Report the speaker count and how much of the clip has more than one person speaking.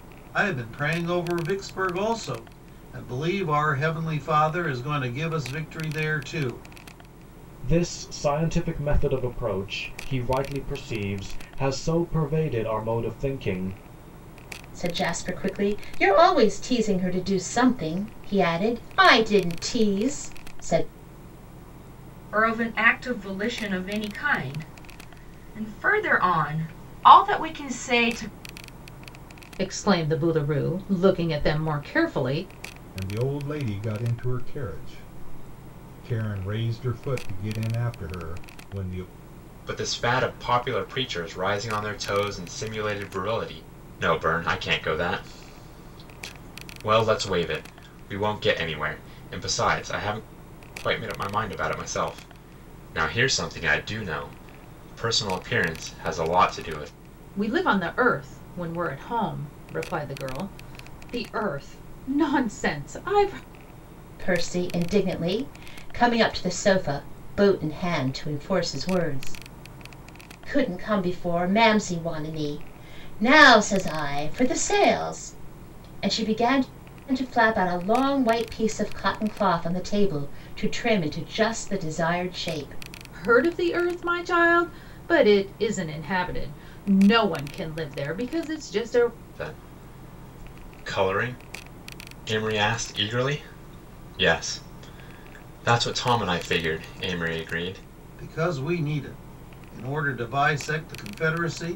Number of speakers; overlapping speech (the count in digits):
7, no overlap